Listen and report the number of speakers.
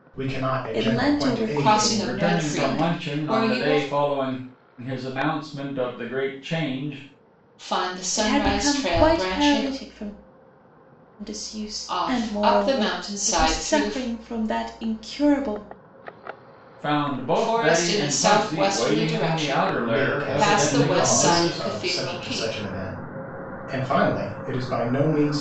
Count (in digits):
4